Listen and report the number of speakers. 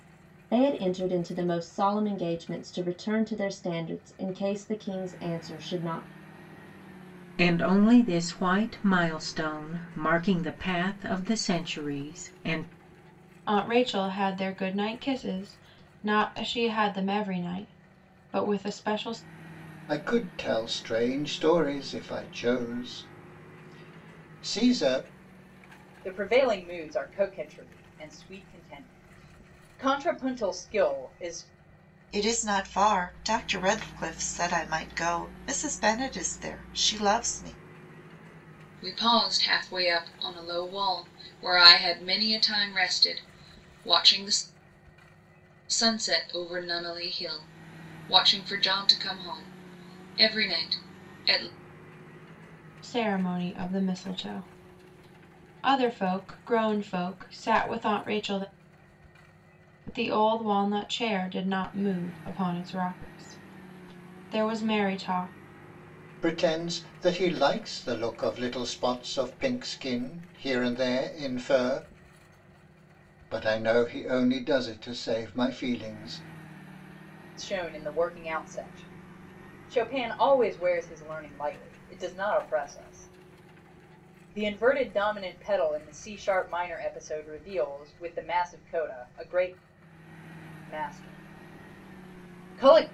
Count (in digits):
7